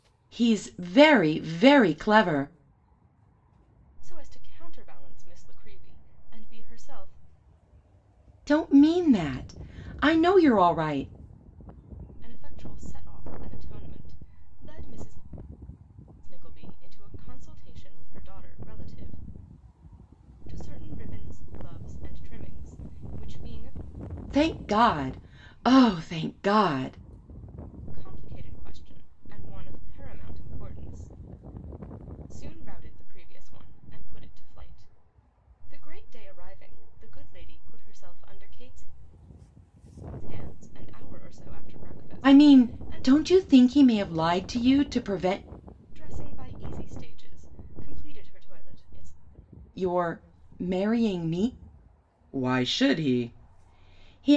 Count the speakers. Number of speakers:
2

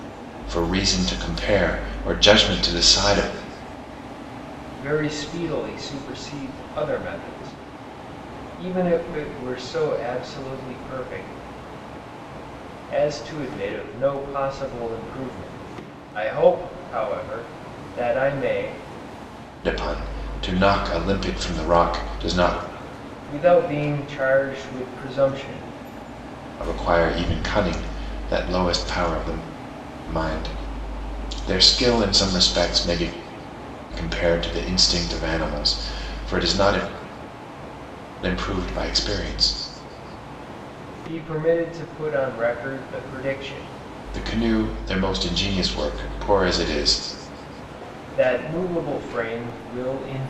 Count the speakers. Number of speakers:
2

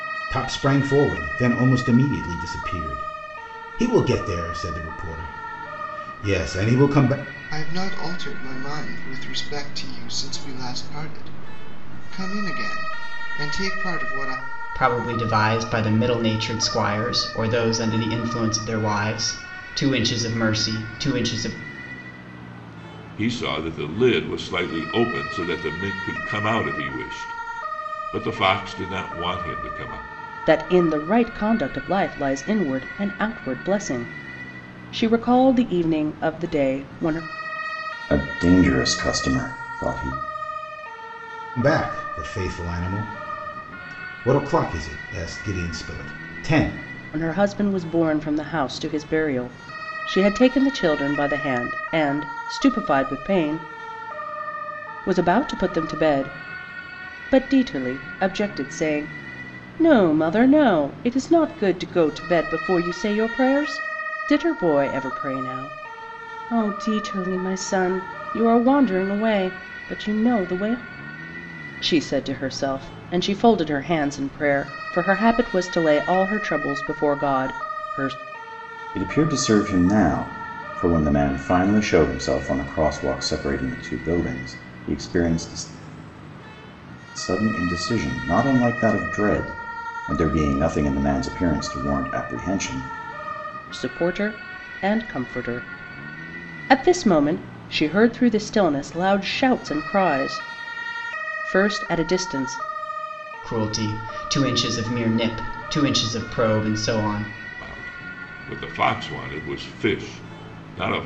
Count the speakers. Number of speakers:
6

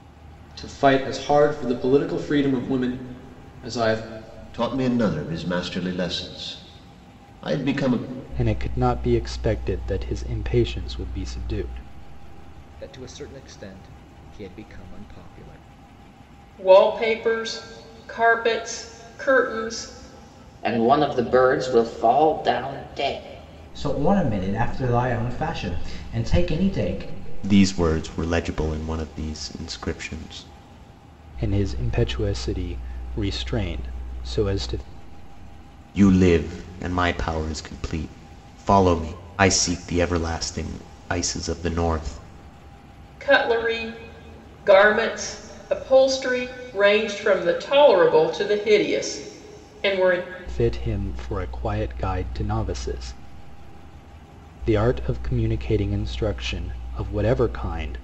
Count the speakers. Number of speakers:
8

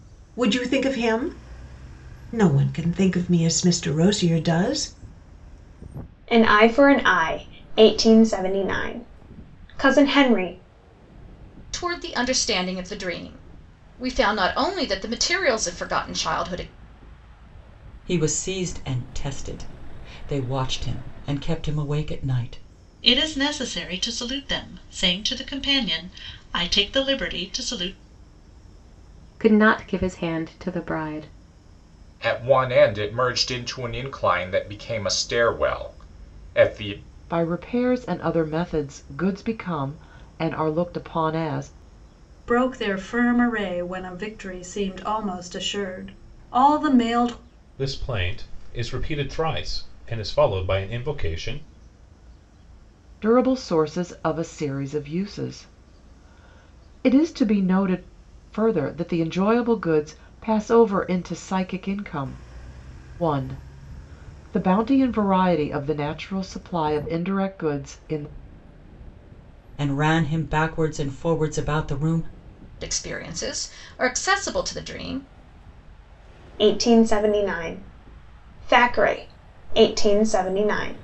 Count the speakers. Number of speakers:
10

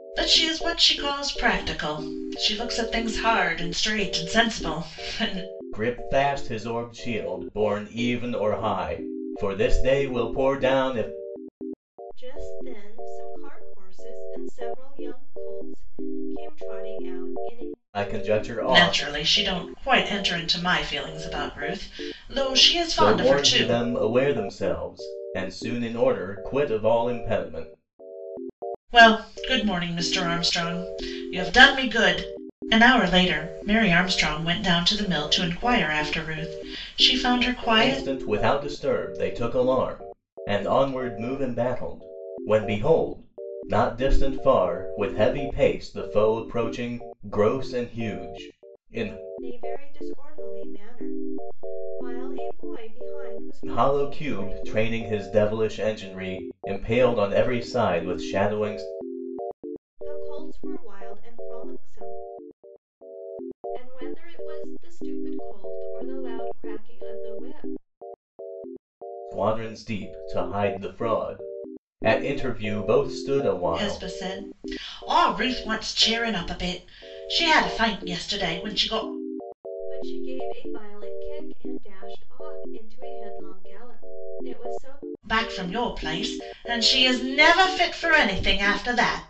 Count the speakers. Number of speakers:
3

